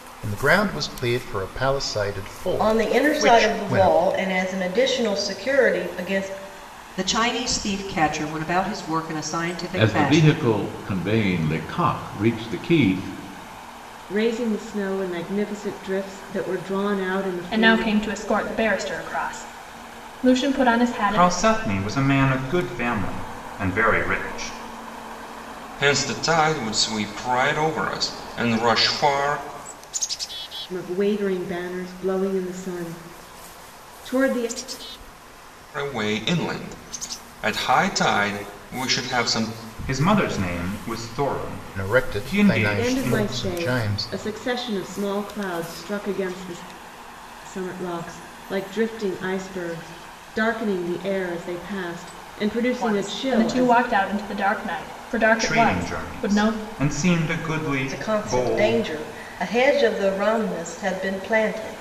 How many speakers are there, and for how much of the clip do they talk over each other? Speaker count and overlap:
8, about 13%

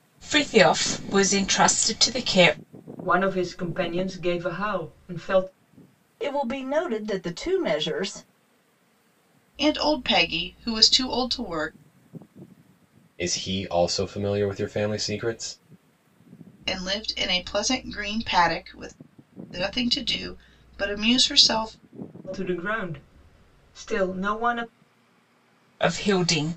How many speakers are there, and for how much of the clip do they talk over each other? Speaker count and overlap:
5, no overlap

